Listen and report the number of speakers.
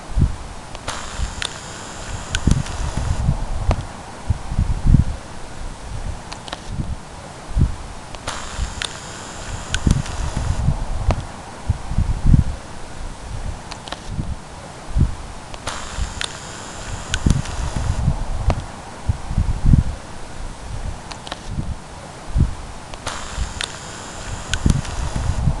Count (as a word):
zero